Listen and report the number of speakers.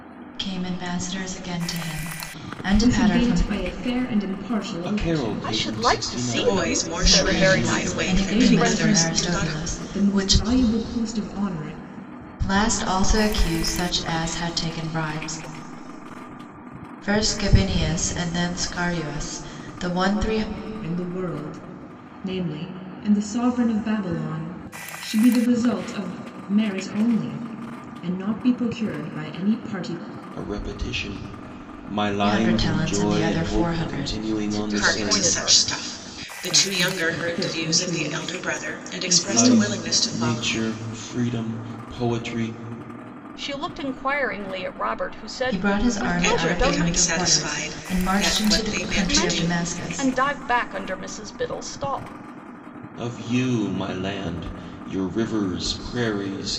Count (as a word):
five